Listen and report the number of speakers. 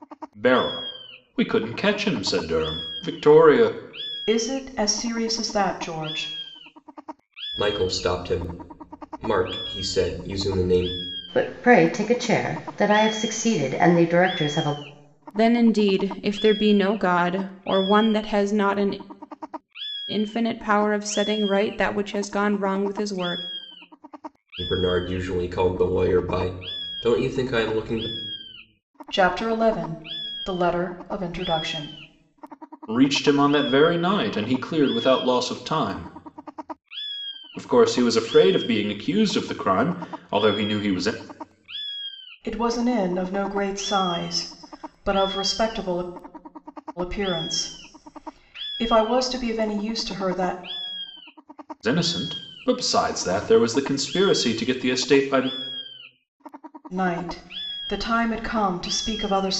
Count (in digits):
5